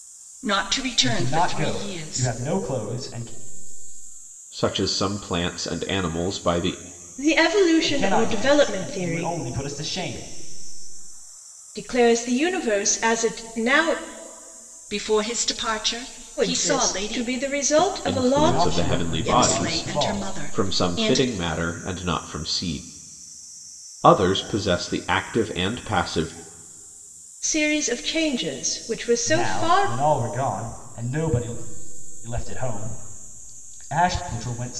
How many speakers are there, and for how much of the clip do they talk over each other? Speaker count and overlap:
4, about 21%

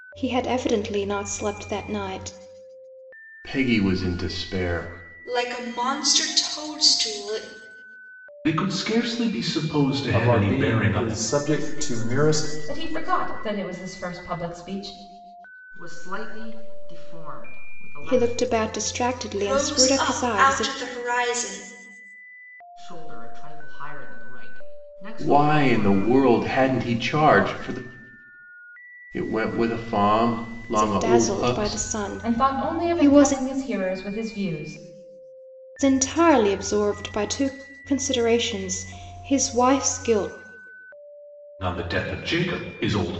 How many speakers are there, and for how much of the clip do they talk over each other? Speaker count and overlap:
7, about 18%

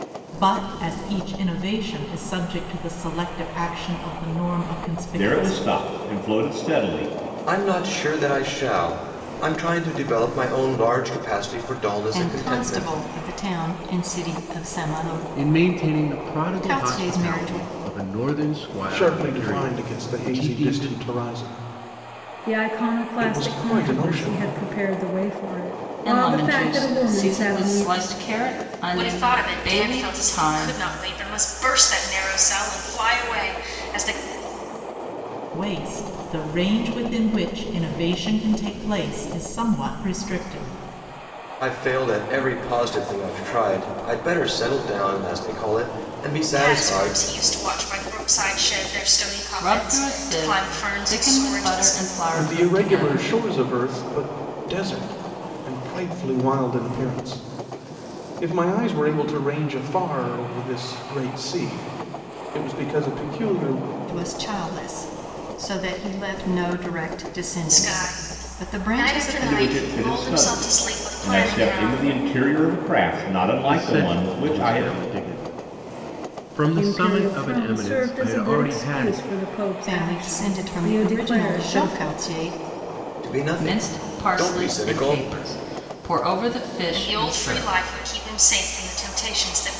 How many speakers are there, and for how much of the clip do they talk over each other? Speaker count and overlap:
9, about 32%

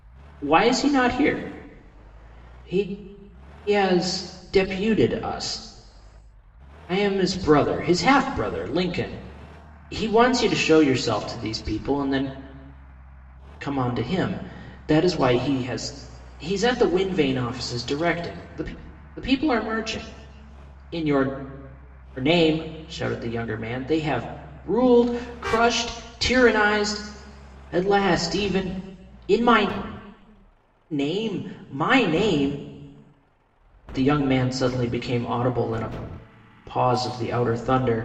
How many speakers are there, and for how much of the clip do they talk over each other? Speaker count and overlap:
1, no overlap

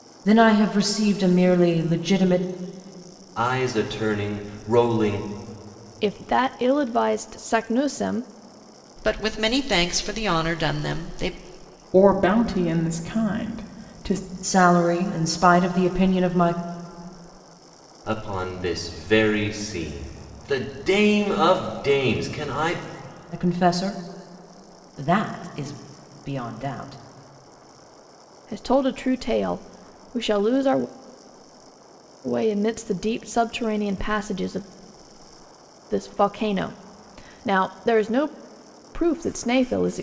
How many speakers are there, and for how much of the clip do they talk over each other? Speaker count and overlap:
5, no overlap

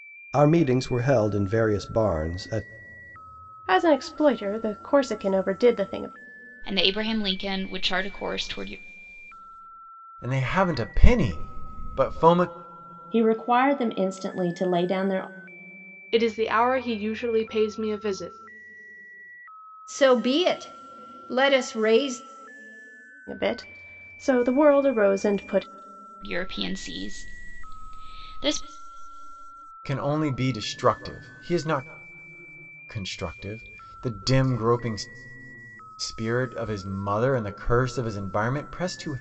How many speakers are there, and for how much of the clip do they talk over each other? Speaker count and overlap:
7, no overlap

